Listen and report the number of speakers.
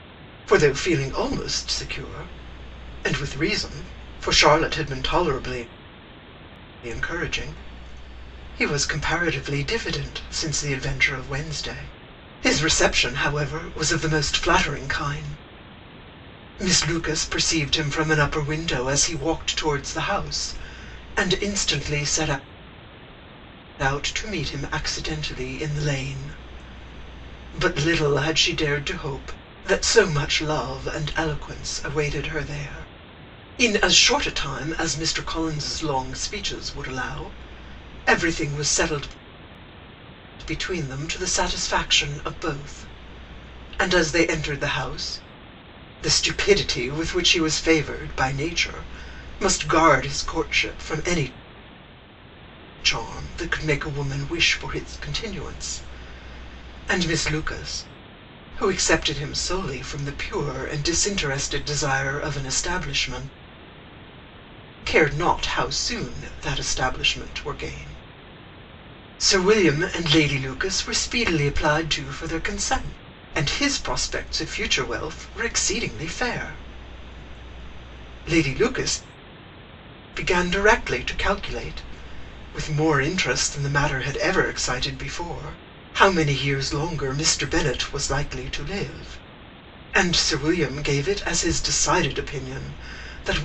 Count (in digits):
1